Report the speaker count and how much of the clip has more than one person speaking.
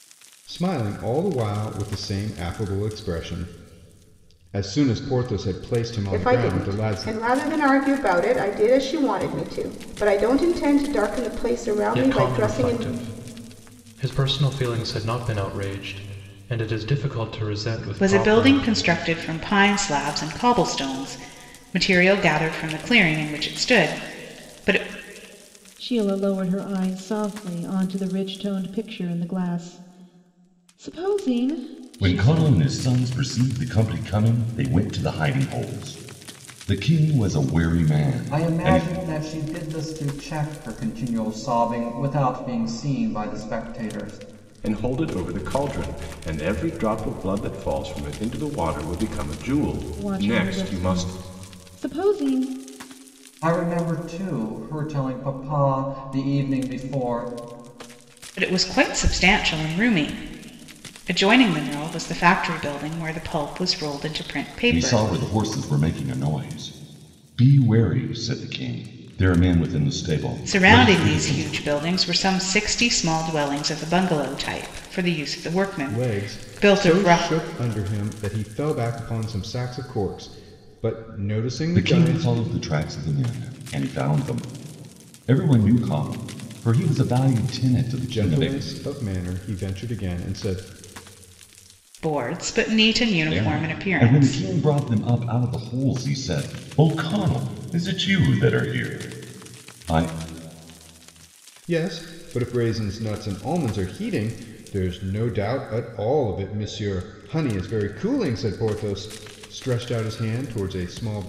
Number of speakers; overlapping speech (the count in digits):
8, about 9%